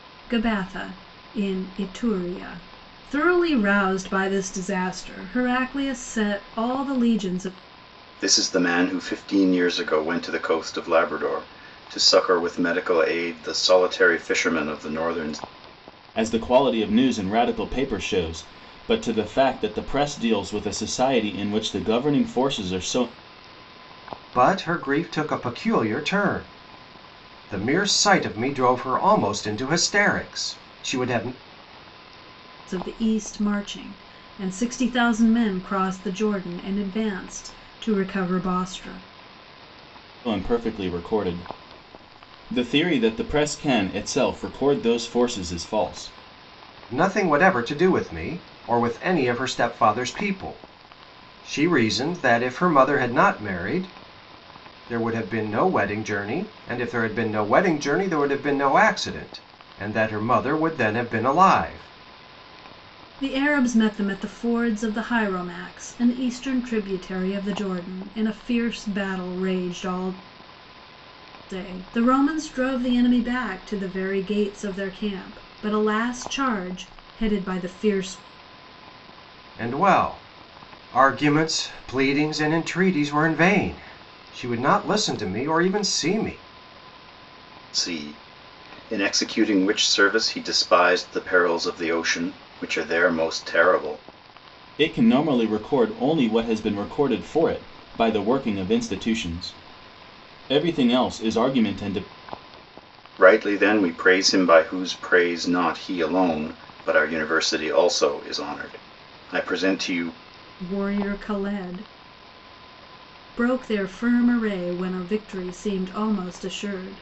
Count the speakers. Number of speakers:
4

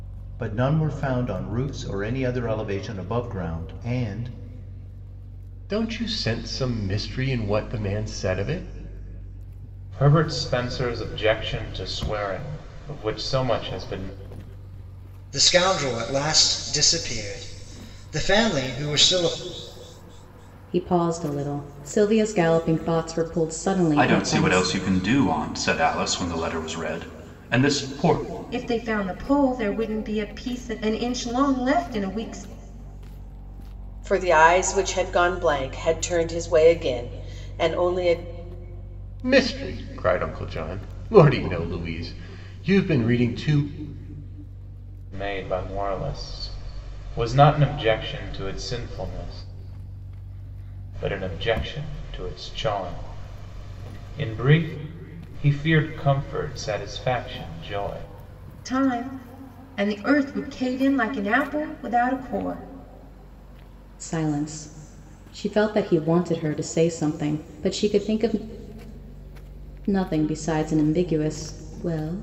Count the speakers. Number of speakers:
8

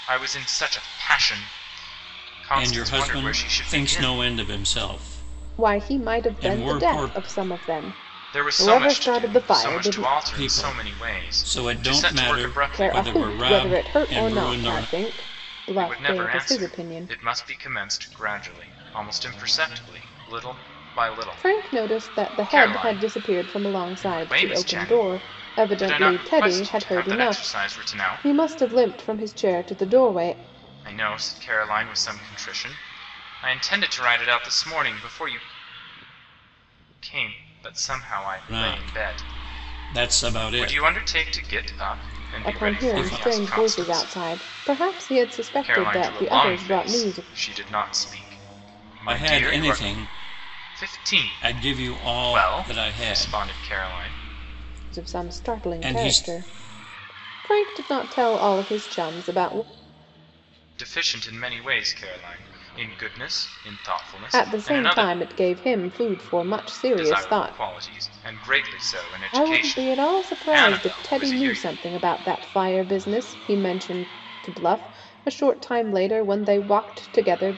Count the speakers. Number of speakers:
3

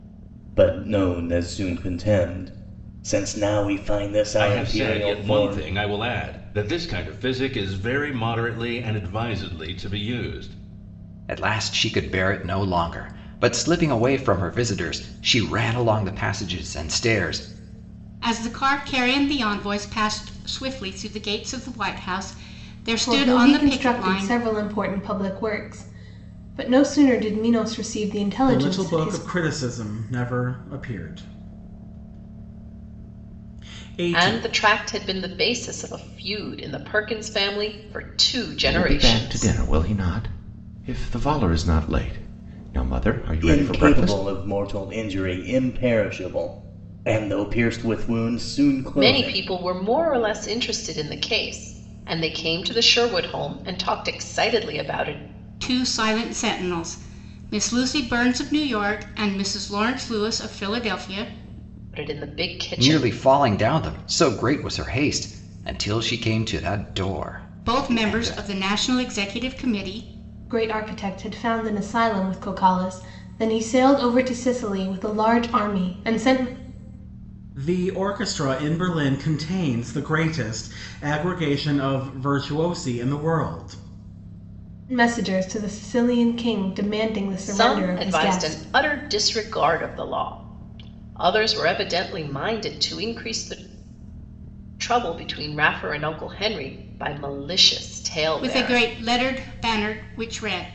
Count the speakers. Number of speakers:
8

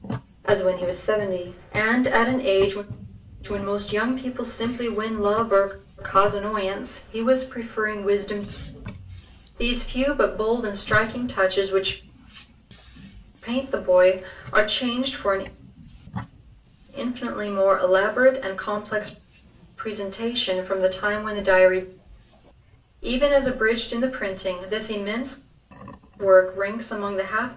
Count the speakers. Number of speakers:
1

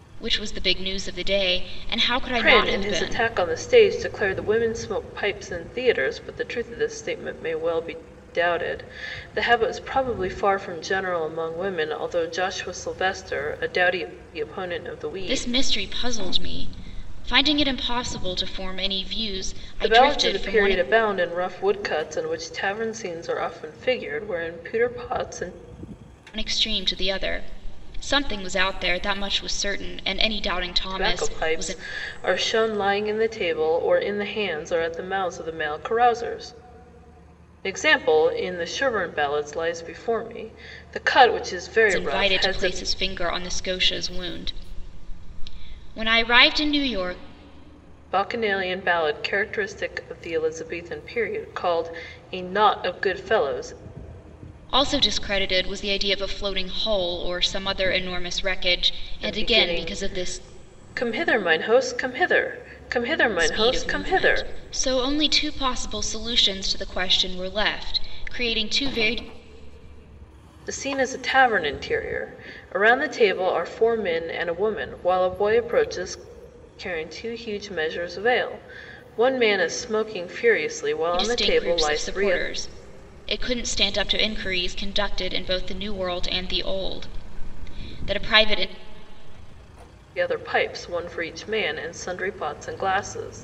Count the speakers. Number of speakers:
2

